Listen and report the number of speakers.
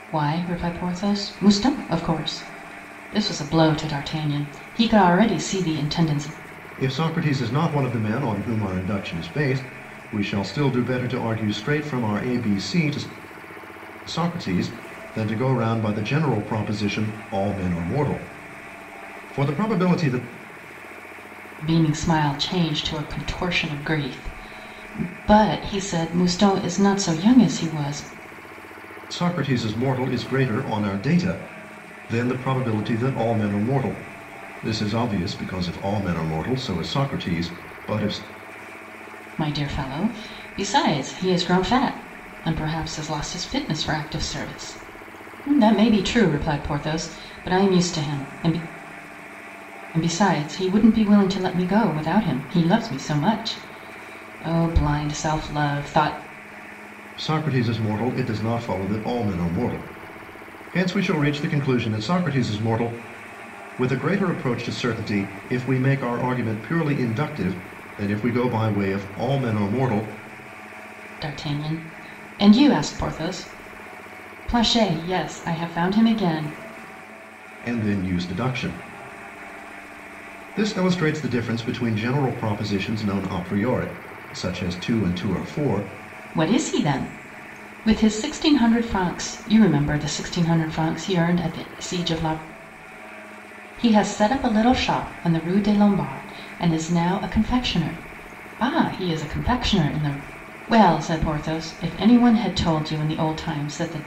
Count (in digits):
2